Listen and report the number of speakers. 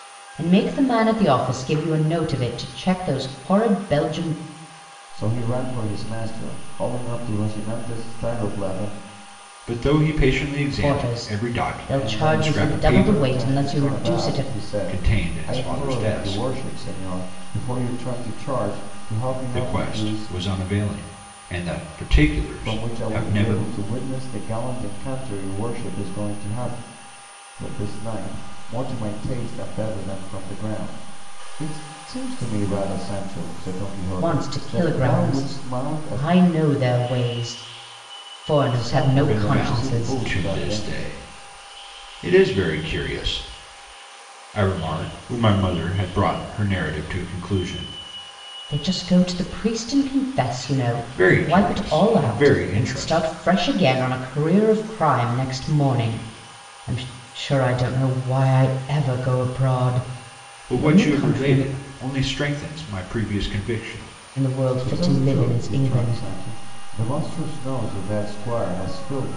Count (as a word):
three